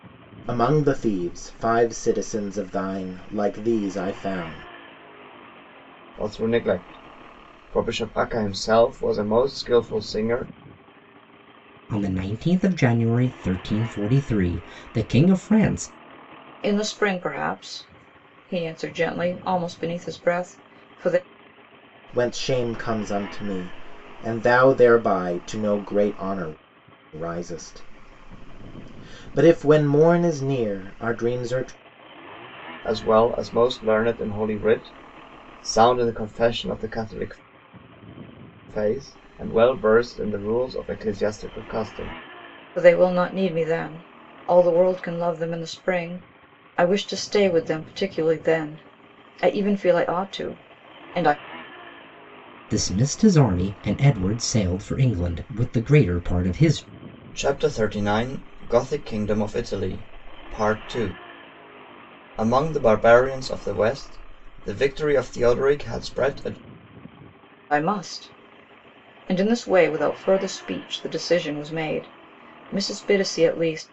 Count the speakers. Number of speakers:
4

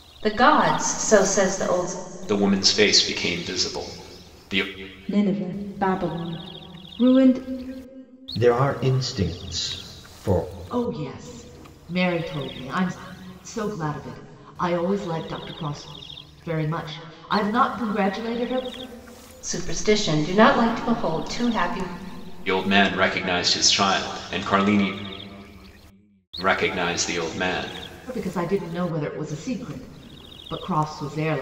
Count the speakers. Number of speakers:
5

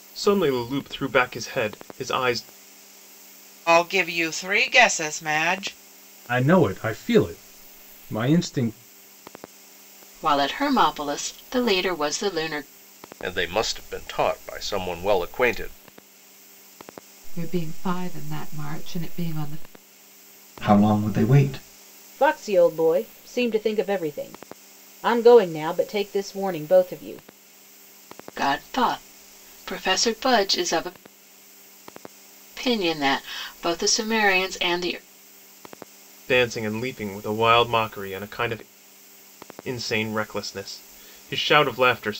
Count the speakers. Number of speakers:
8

